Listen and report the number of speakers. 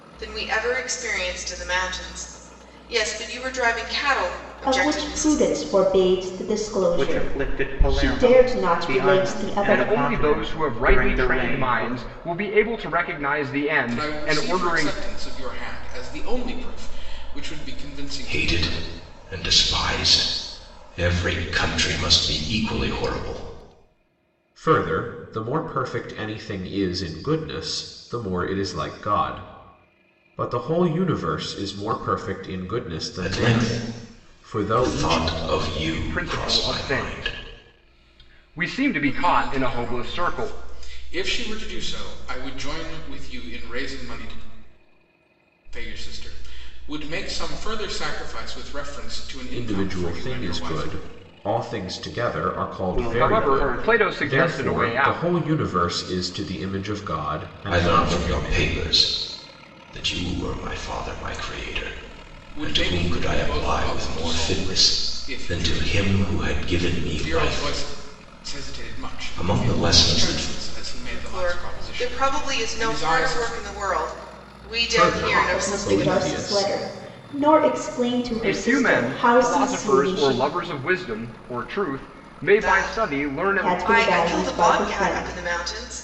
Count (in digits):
7